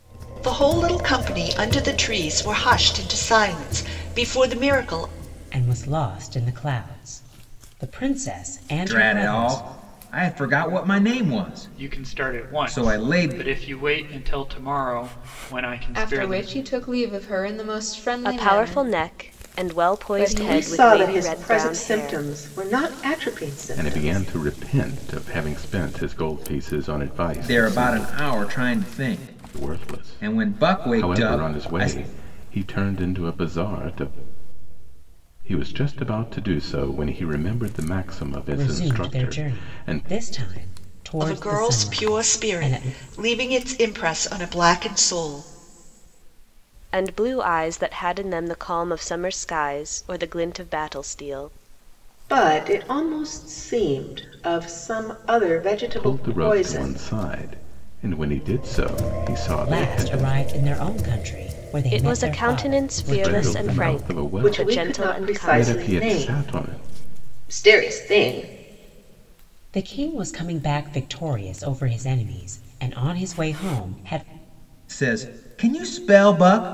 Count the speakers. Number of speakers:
eight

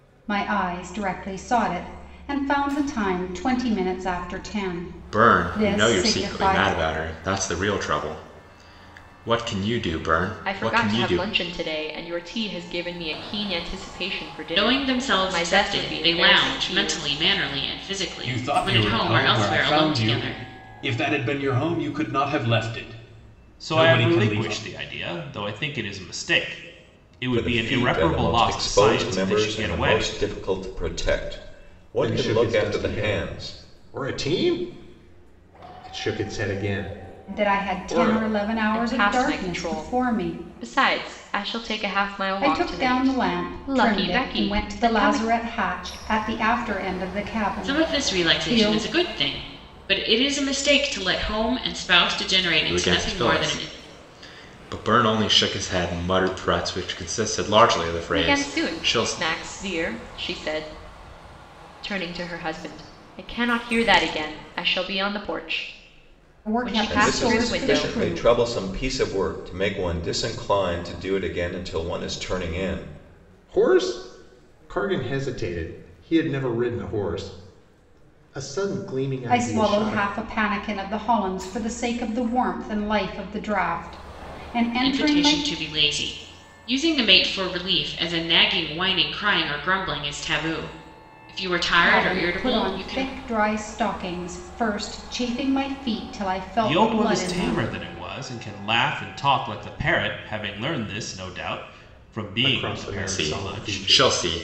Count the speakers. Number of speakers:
eight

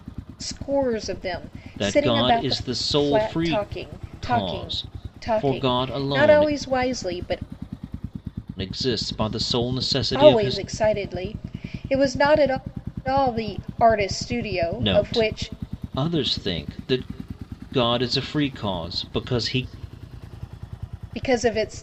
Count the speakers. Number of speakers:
two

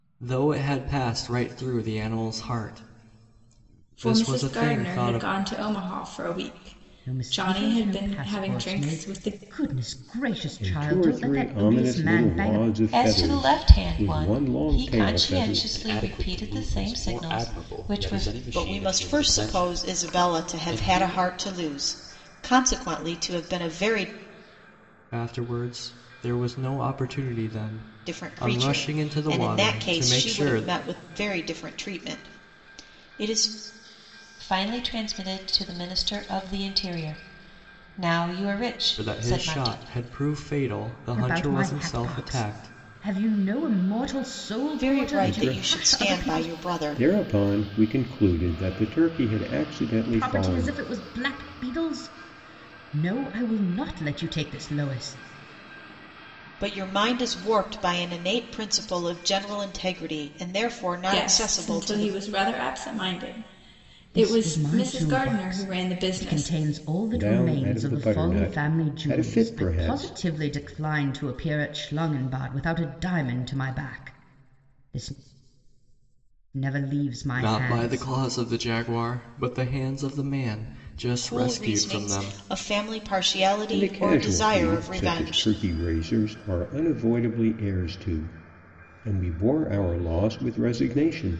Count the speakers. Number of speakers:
seven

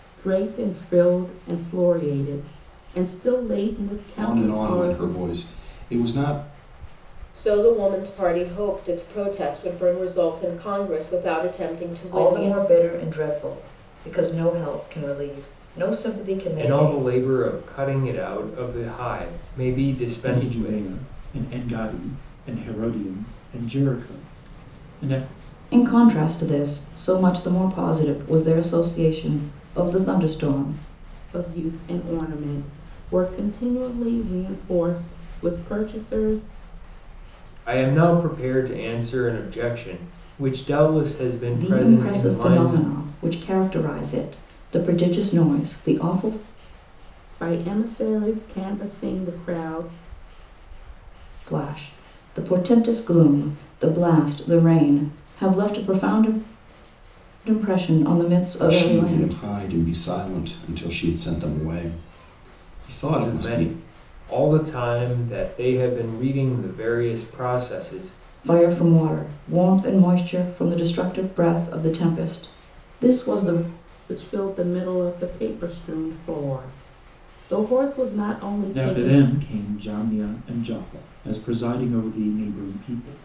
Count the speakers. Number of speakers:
six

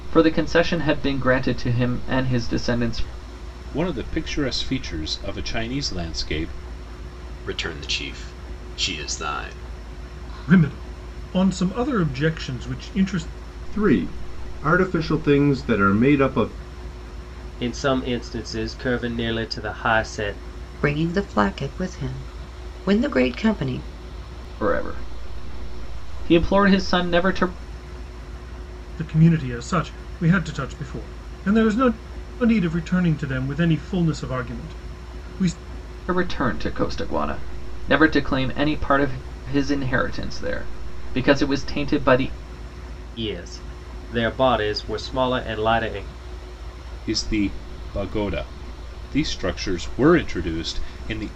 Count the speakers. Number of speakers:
seven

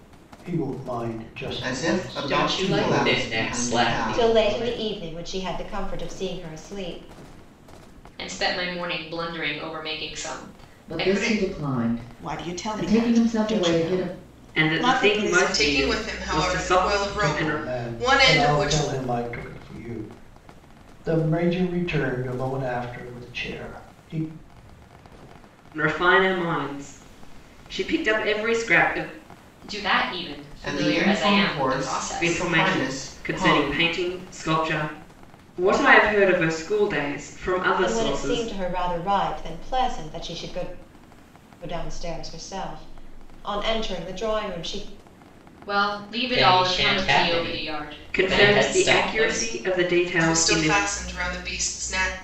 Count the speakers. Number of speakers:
nine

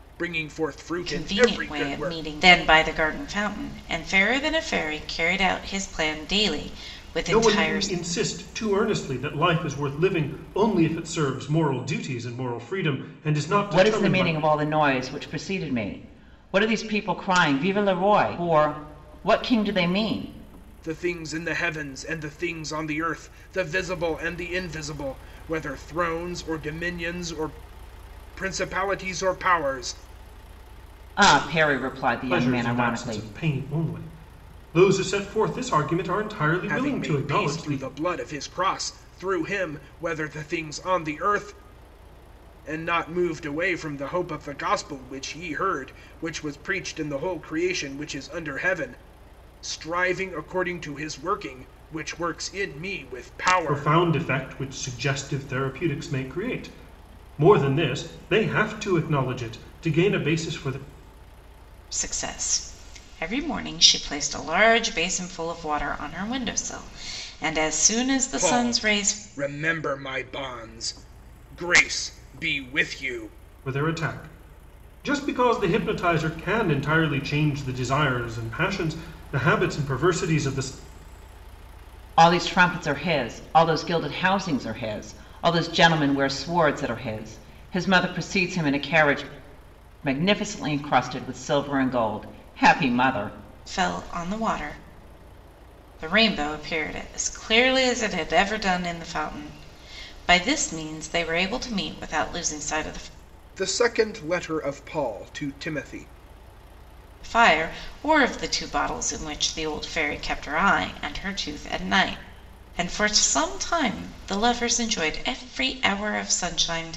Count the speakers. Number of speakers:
four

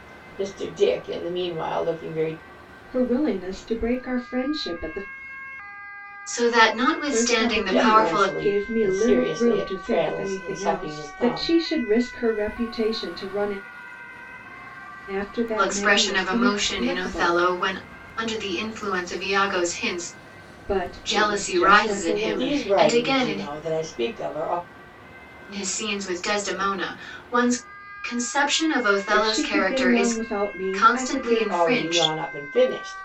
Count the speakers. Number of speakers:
three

